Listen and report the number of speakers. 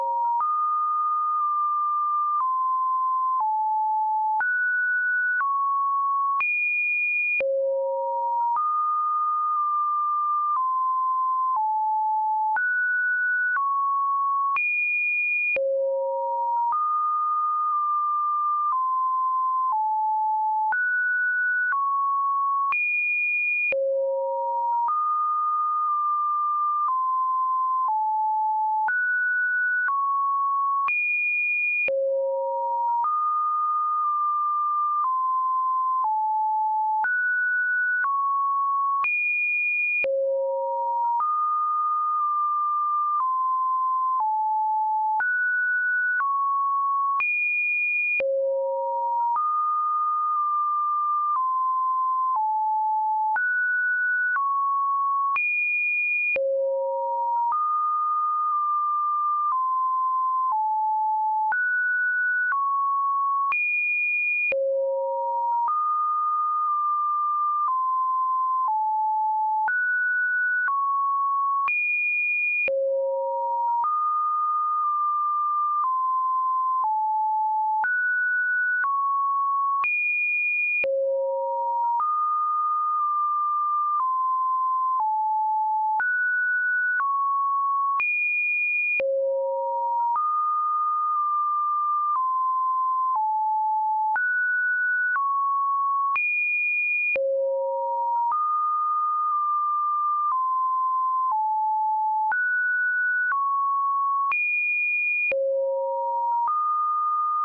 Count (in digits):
0